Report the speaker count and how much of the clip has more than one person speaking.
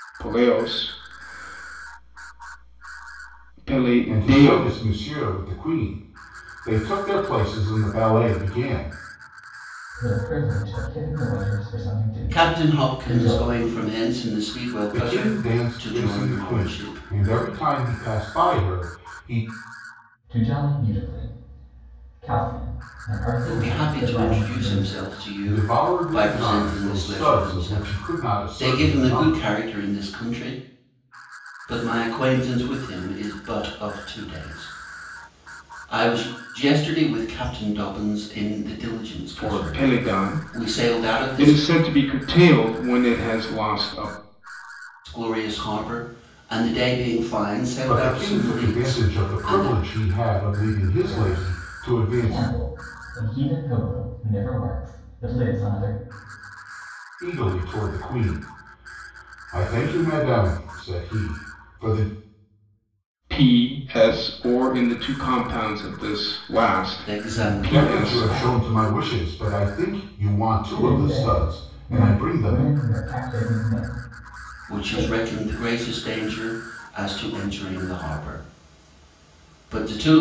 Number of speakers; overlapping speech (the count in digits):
4, about 24%